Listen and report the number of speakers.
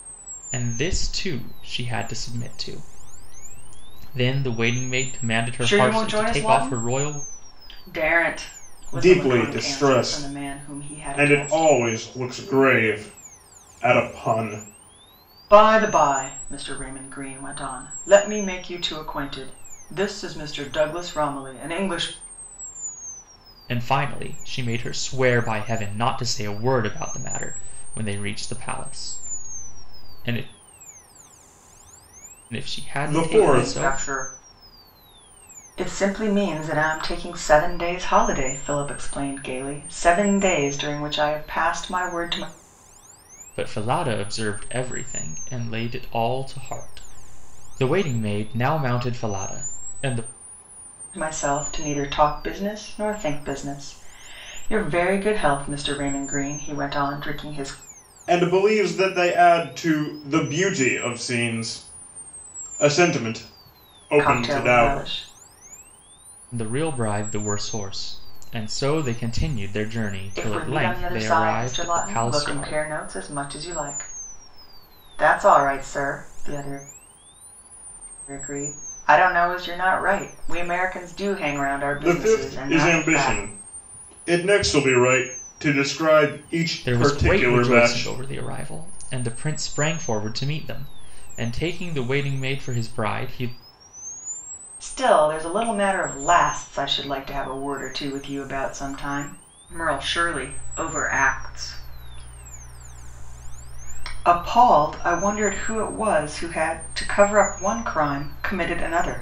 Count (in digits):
3